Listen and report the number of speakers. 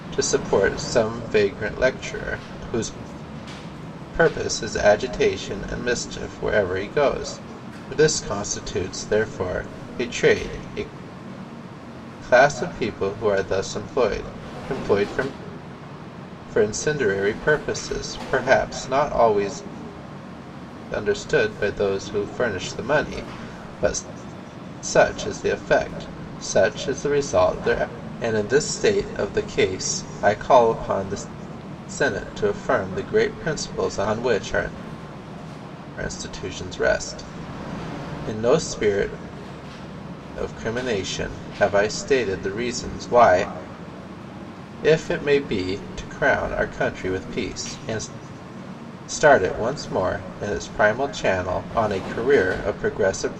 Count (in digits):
1